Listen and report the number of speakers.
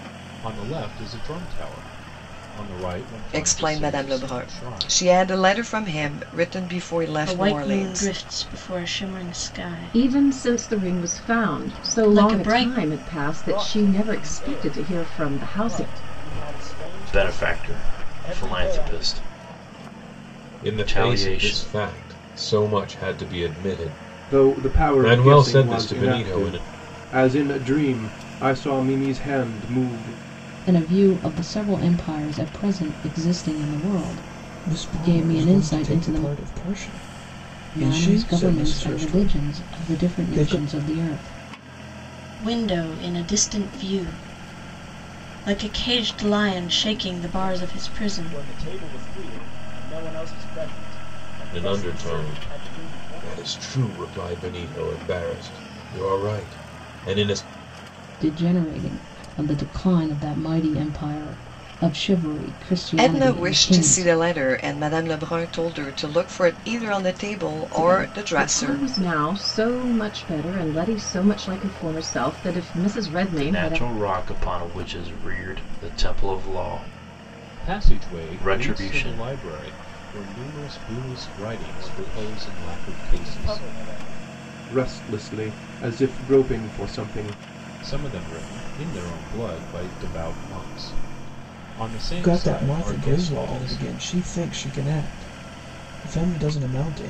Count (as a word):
ten